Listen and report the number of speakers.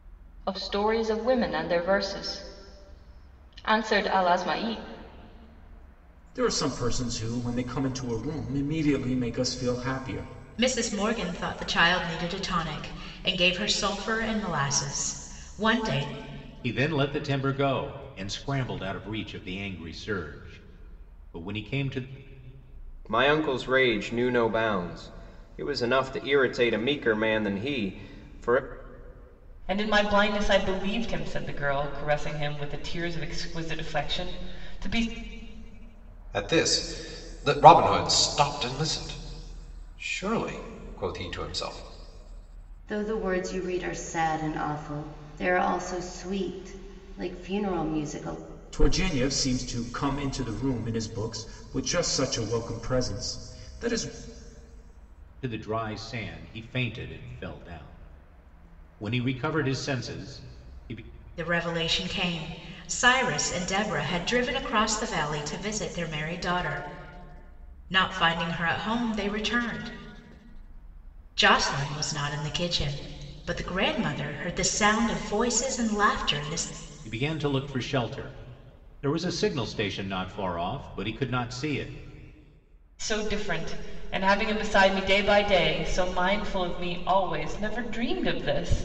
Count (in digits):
8